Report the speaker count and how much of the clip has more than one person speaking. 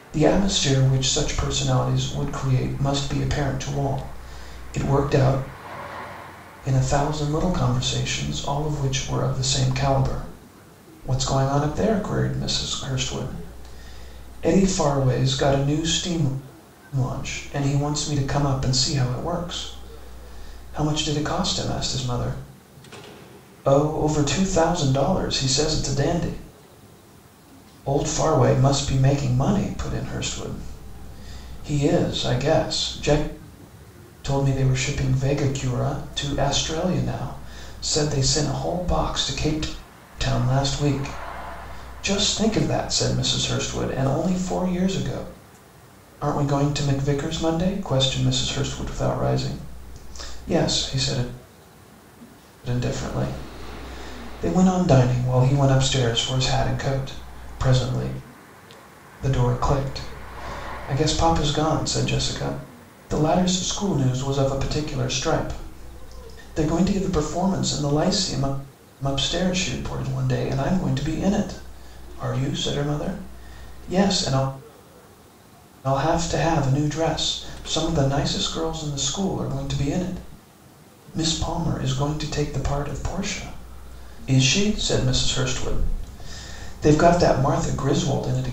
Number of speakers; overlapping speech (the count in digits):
1, no overlap